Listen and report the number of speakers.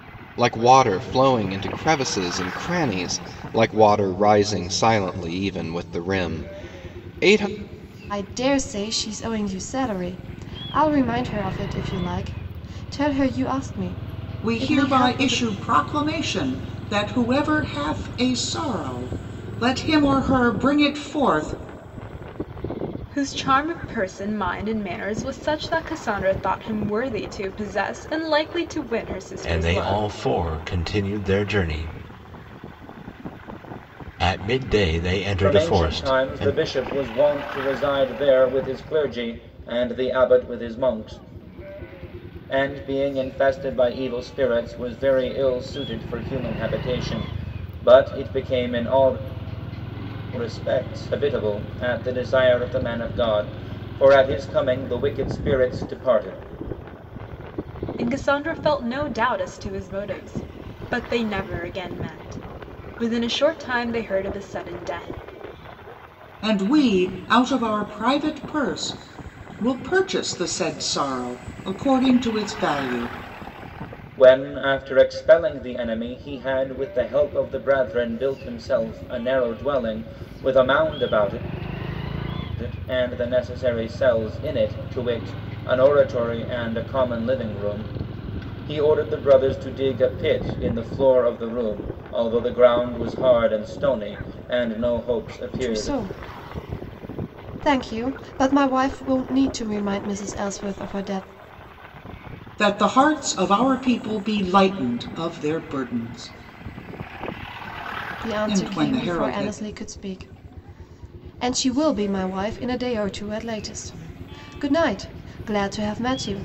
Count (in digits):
6